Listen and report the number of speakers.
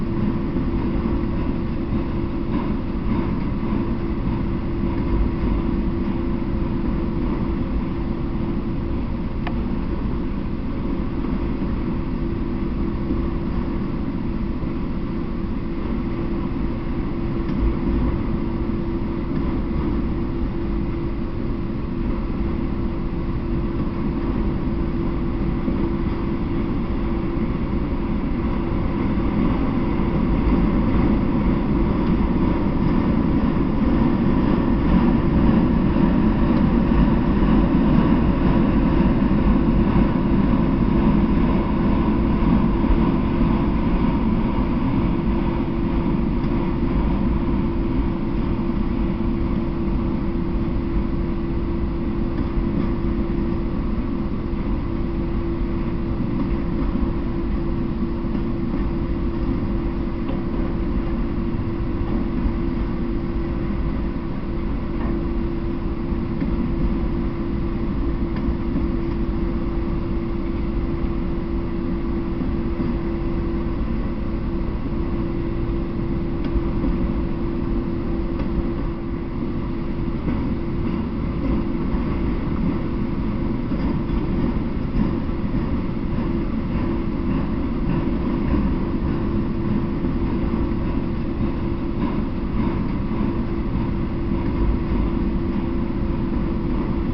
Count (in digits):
0